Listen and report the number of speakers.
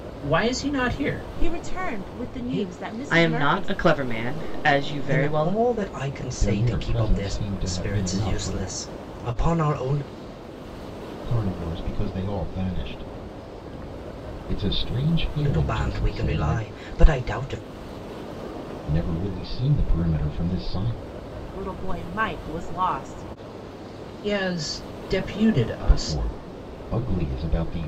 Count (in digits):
5